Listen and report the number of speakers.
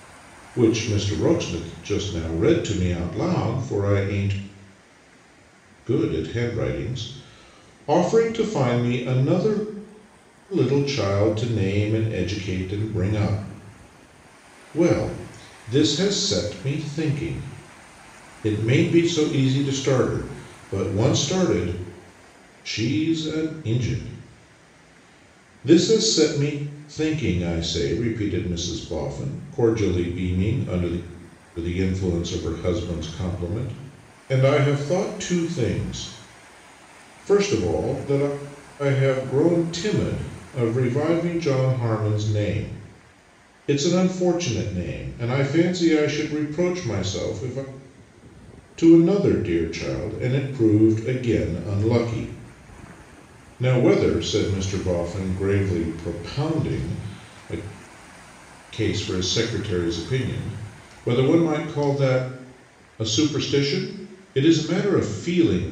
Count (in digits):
1